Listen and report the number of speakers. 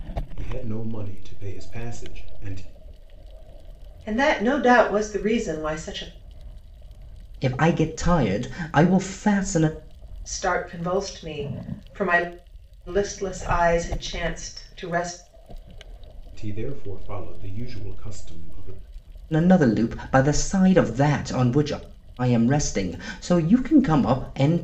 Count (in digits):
3